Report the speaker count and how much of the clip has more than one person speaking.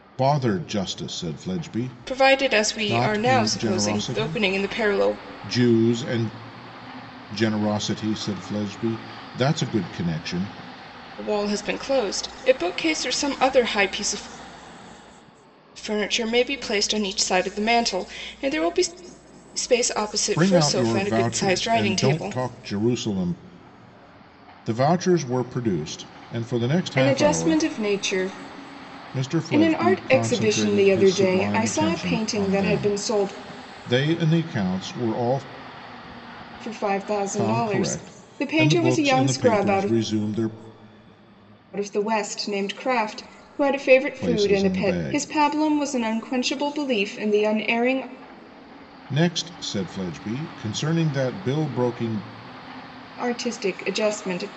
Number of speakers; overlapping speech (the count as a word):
two, about 26%